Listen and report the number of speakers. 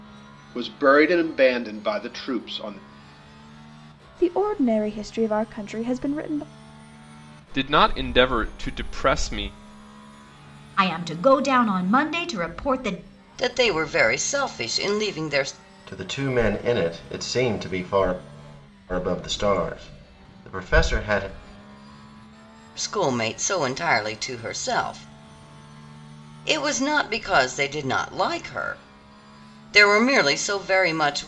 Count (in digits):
6